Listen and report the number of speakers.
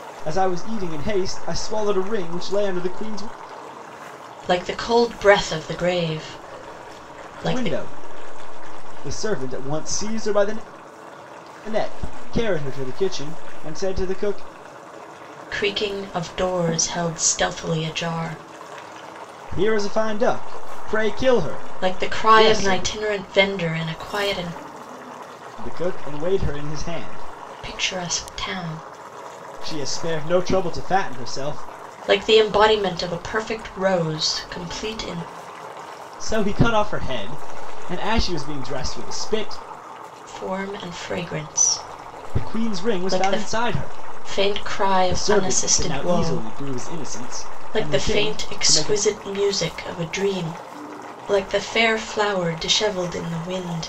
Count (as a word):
two